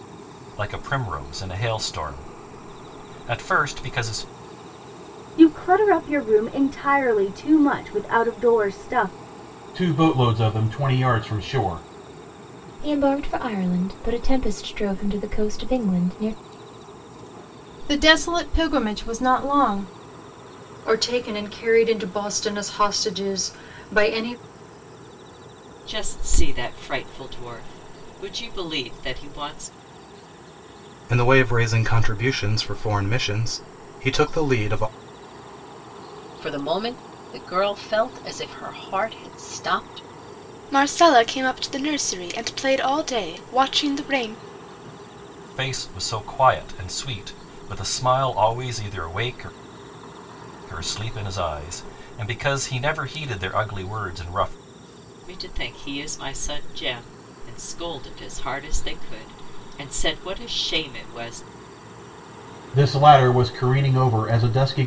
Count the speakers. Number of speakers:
10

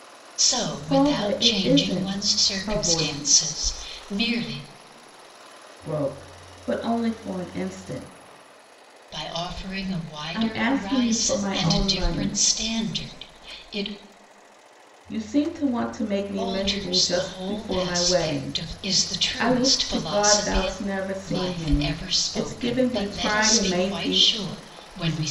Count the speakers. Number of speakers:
2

